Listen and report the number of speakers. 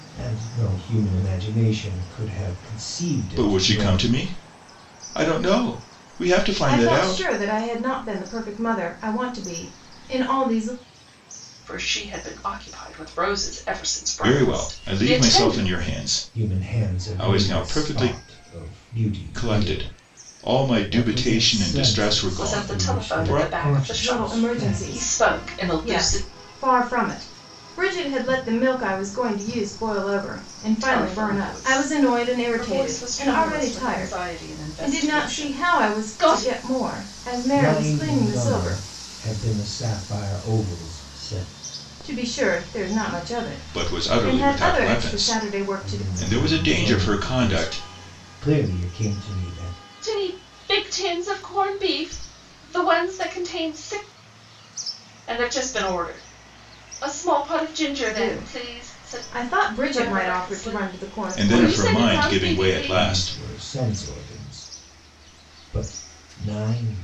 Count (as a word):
four